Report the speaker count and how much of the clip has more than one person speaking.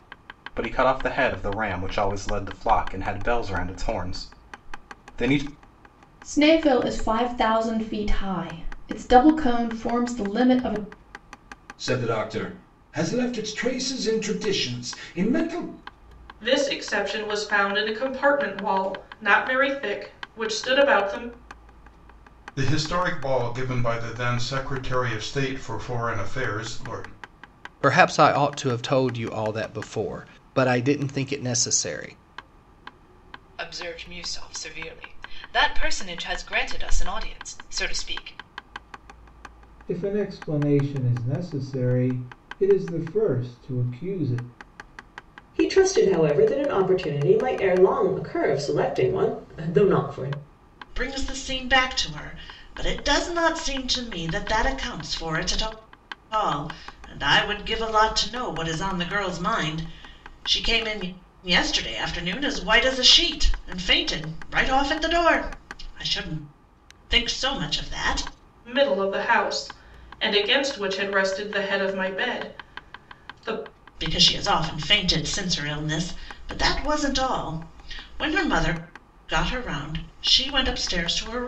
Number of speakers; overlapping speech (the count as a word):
ten, no overlap